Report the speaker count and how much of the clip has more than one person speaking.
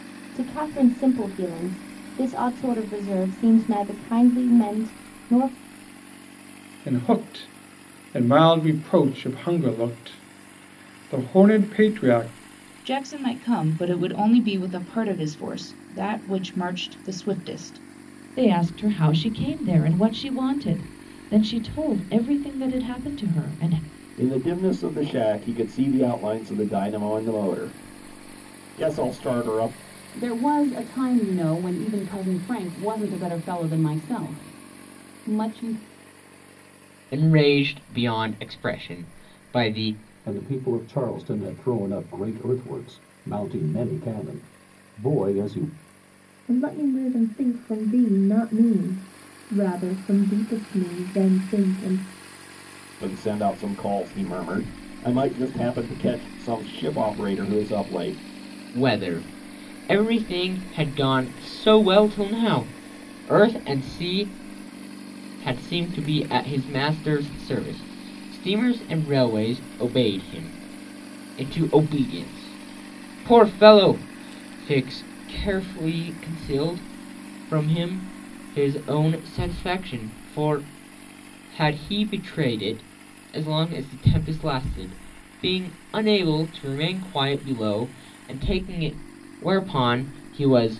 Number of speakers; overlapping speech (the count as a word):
nine, no overlap